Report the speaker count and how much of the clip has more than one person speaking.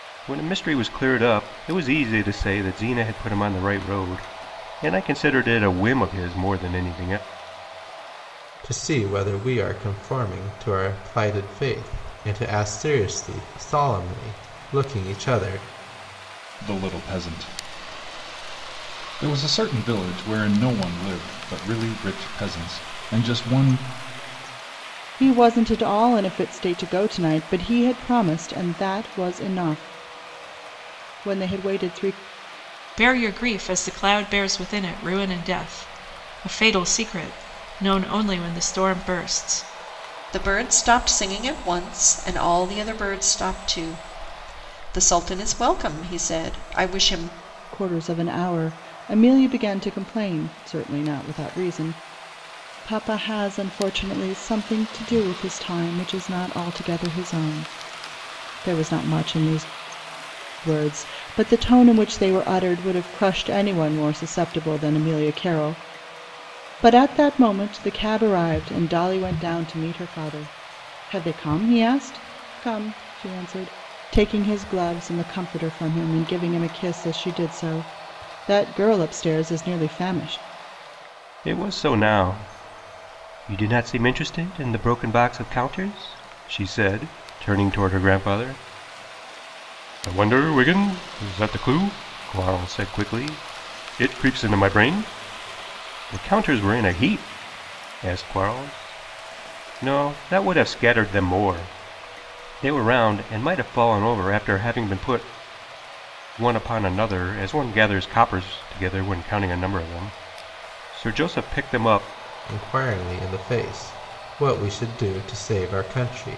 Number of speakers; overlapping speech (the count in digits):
6, no overlap